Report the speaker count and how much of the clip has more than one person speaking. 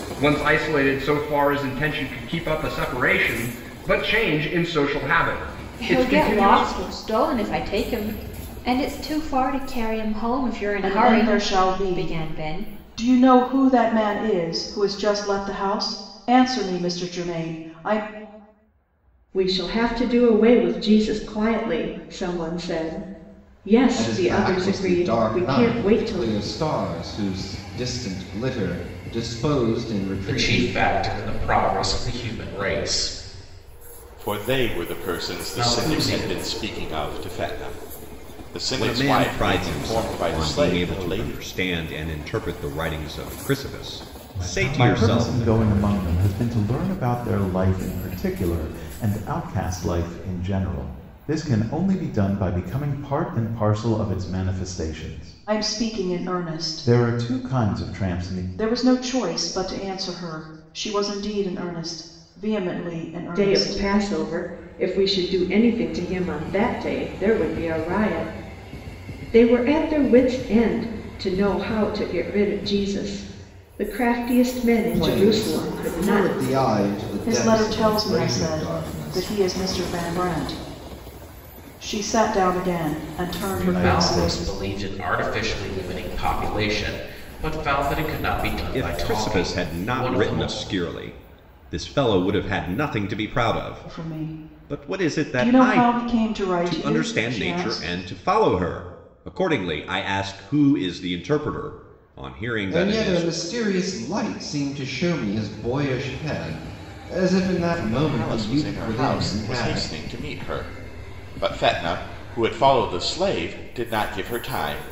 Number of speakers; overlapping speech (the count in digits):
10, about 26%